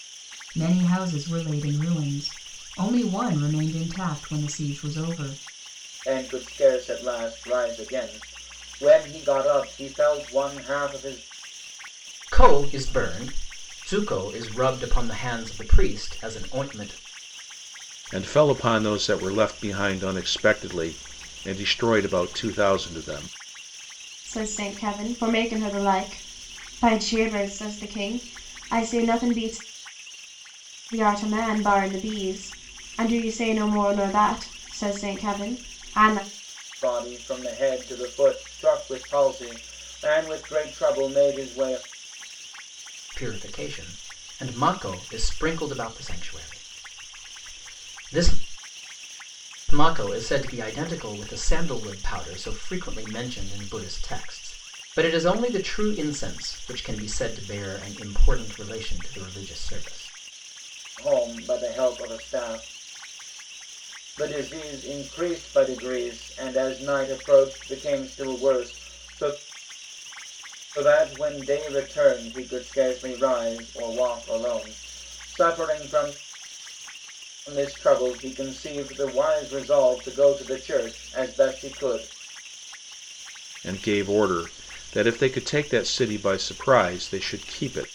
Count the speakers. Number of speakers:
five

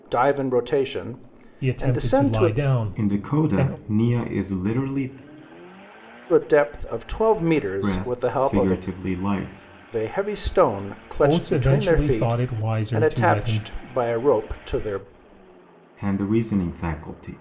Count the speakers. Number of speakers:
three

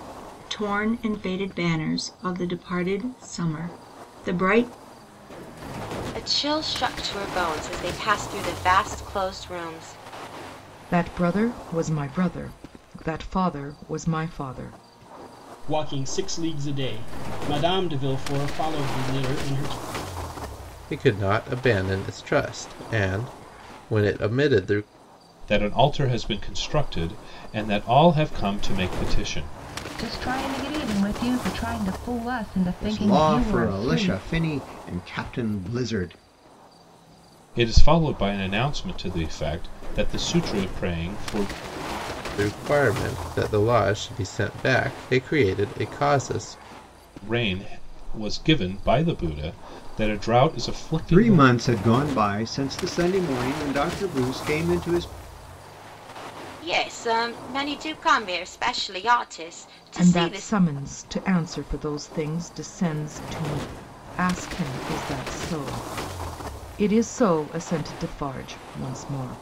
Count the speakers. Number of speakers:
eight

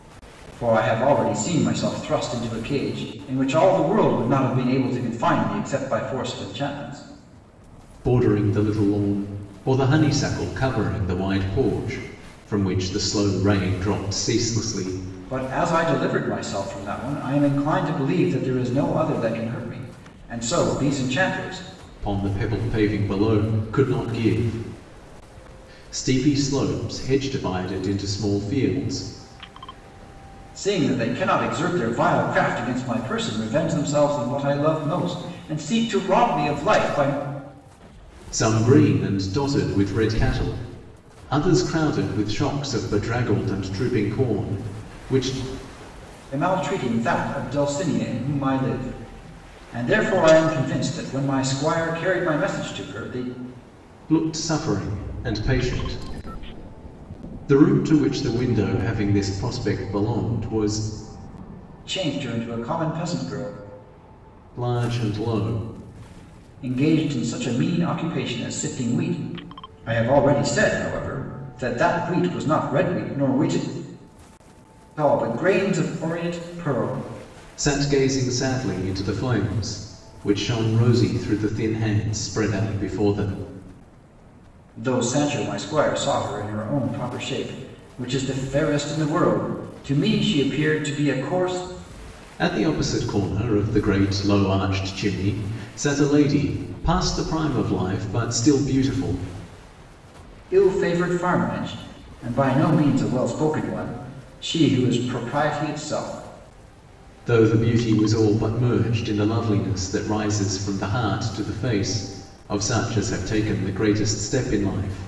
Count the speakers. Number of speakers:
two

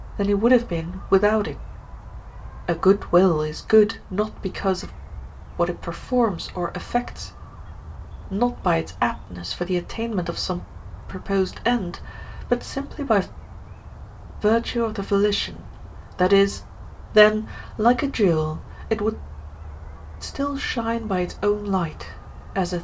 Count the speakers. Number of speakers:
one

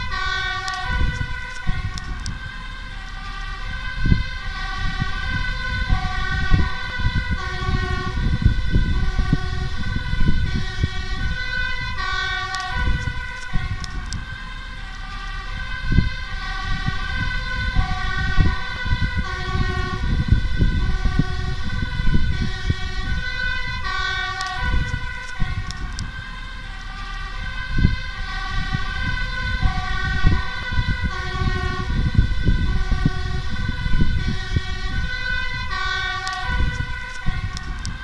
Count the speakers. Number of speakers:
zero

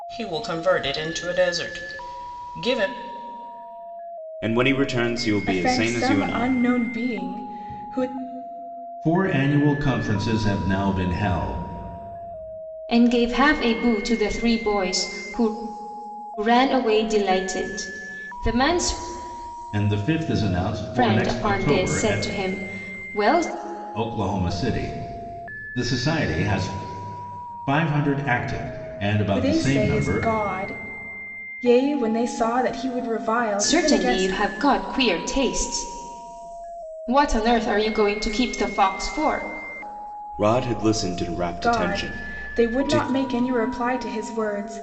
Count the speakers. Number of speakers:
five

